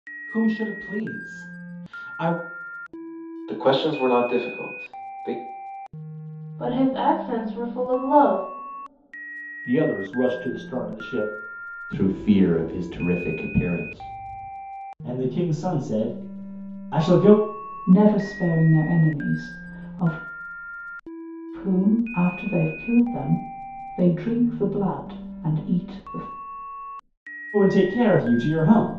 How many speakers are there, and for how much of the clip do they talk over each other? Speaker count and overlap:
7, no overlap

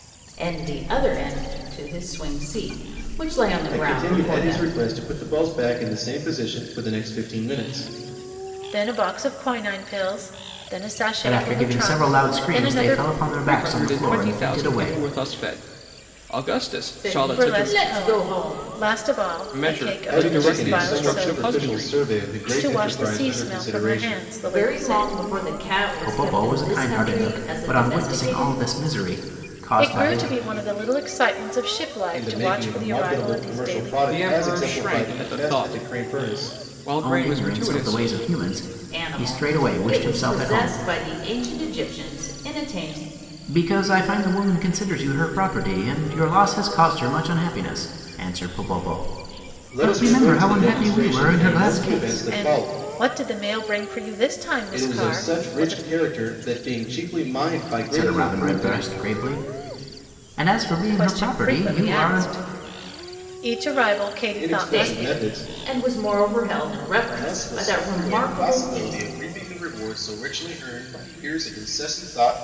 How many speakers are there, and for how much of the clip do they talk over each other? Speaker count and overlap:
5, about 44%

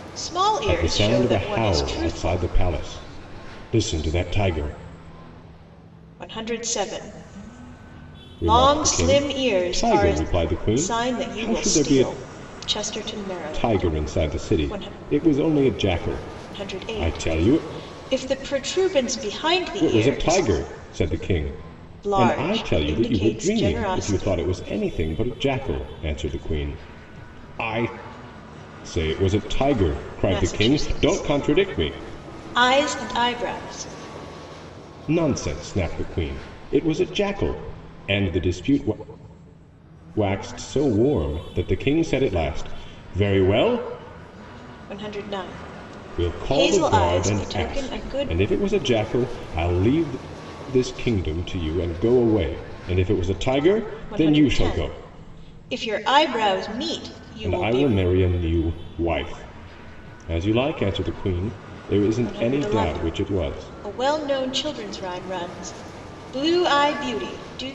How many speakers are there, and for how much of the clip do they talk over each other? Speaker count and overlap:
2, about 26%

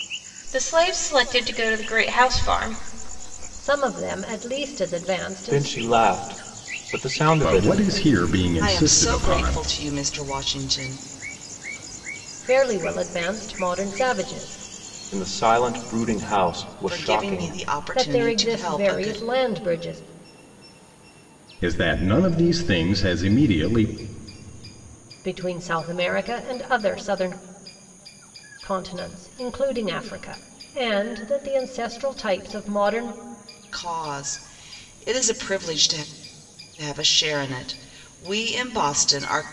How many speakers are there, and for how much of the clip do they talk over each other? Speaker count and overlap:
5, about 10%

